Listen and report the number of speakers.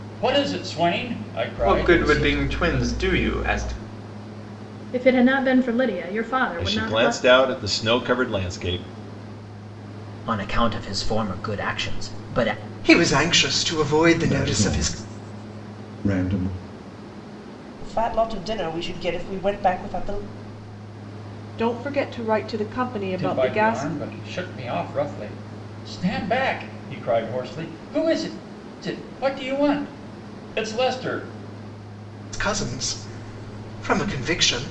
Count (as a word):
nine